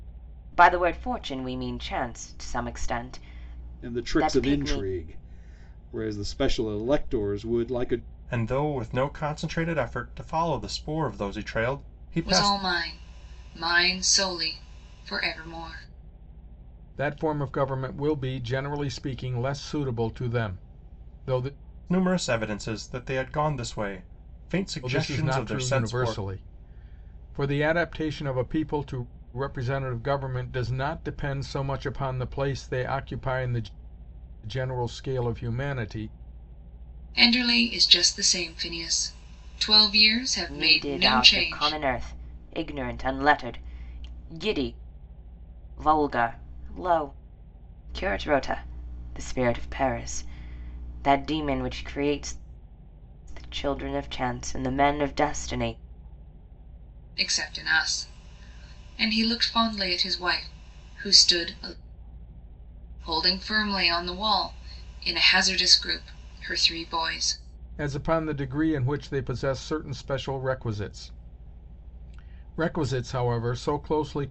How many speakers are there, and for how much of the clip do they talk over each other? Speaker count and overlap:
five, about 6%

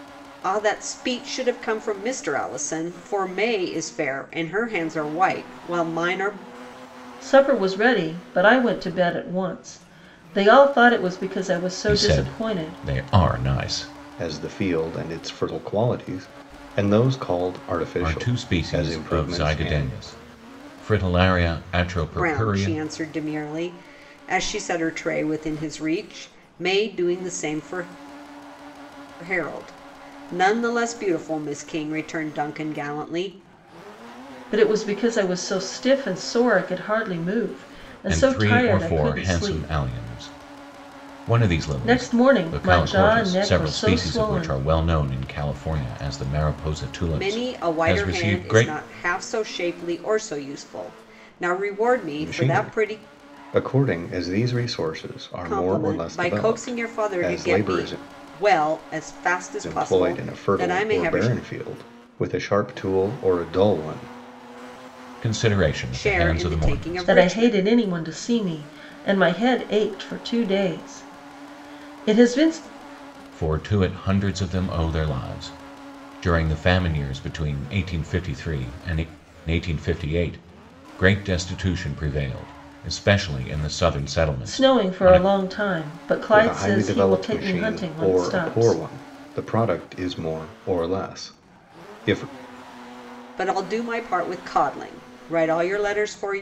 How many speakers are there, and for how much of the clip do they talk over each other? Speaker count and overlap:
four, about 21%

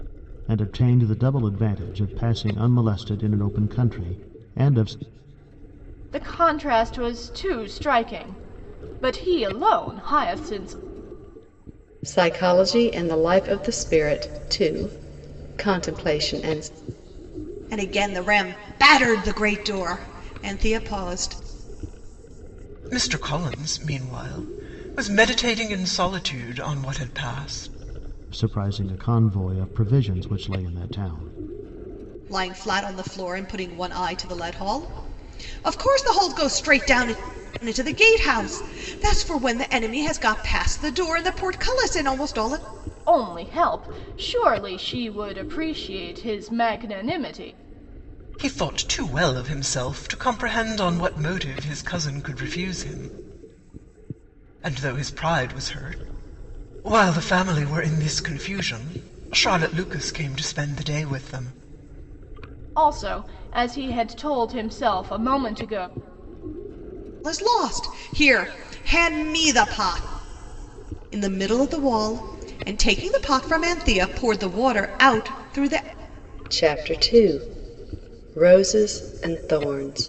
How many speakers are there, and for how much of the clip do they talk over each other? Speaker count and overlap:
five, no overlap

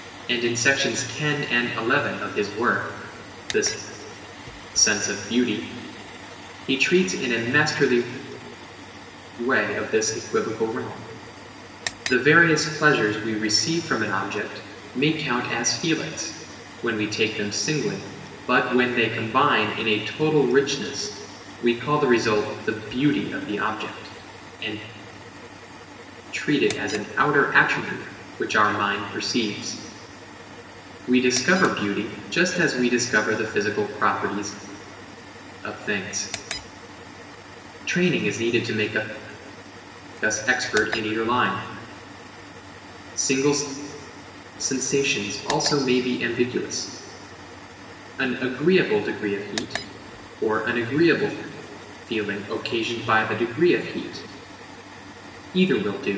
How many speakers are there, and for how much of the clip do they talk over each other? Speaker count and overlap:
one, no overlap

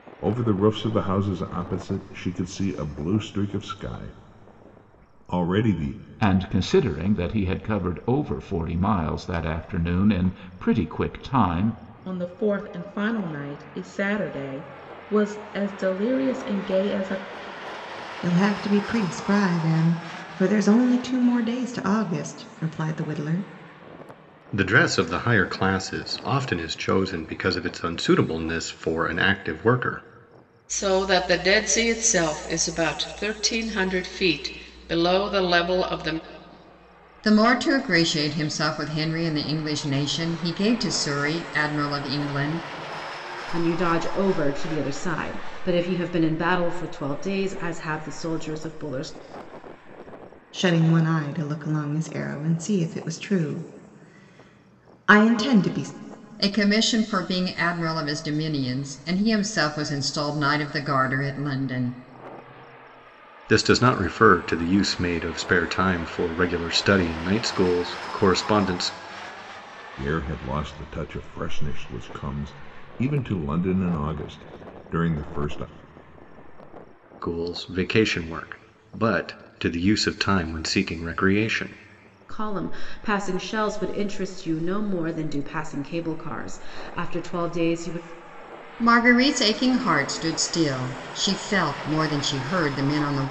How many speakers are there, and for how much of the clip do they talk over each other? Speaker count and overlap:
eight, no overlap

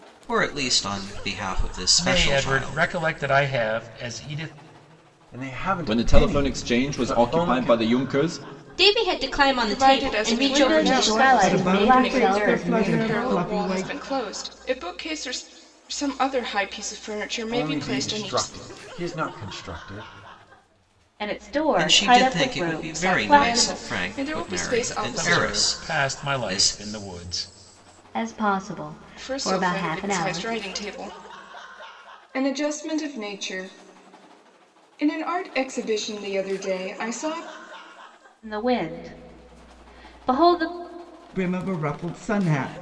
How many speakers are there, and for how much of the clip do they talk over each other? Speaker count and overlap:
nine, about 34%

